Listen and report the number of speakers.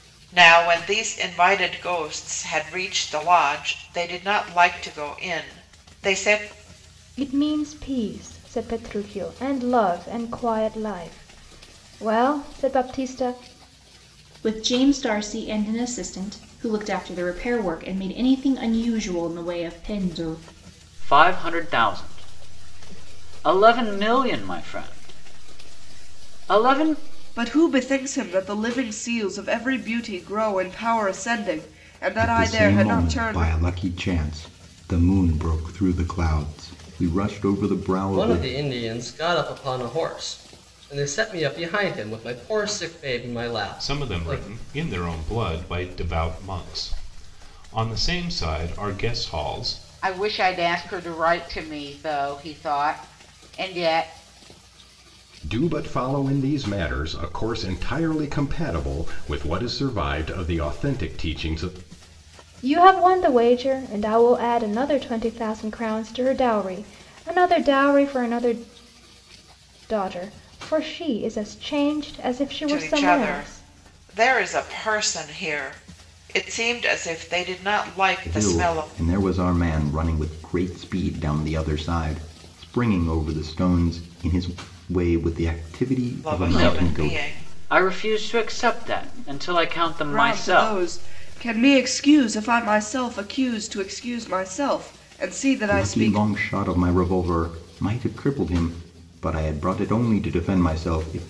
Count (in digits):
10